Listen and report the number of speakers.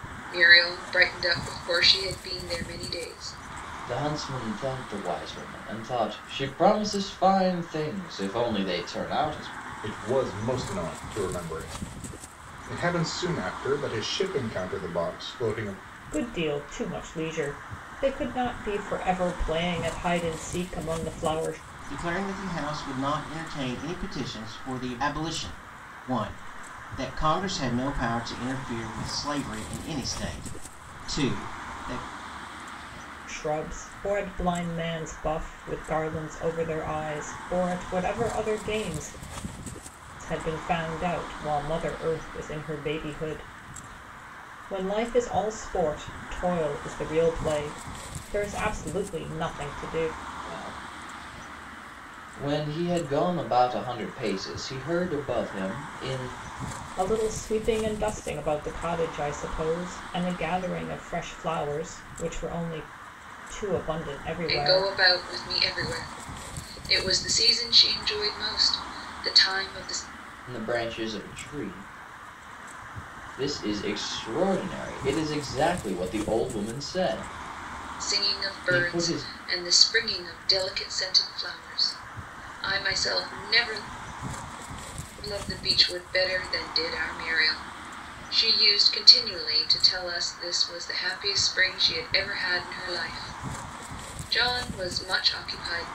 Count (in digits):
5